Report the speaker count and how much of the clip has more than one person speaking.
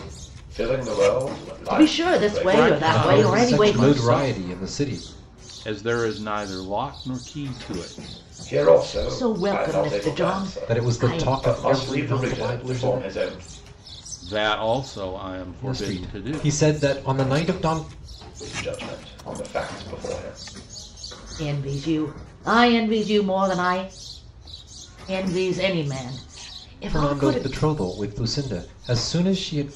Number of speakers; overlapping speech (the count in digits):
4, about 28%